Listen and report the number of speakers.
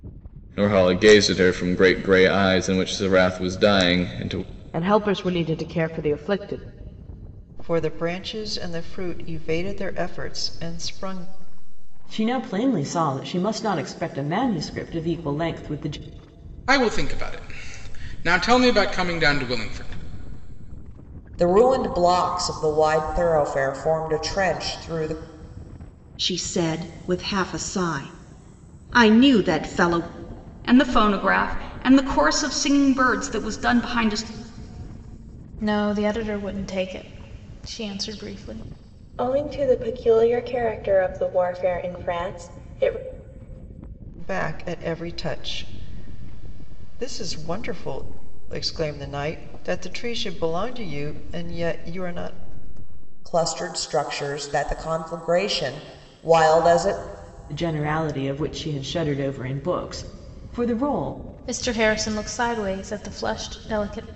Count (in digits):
10